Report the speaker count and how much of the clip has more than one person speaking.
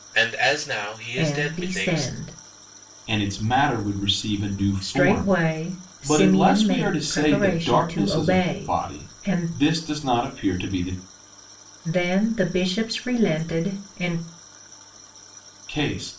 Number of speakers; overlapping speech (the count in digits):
3, about 30%